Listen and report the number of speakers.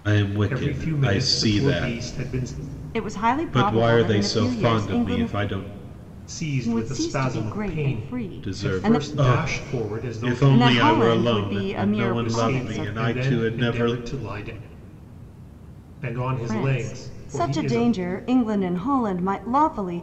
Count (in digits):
3